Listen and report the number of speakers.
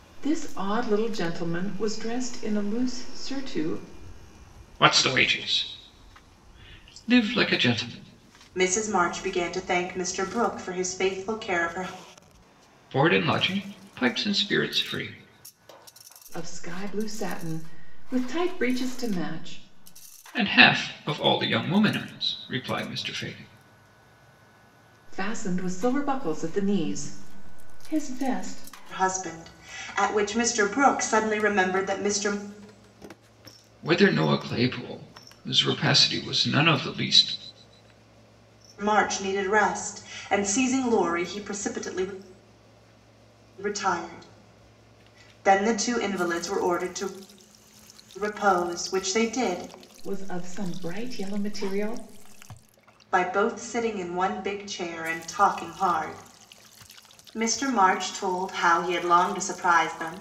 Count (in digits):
3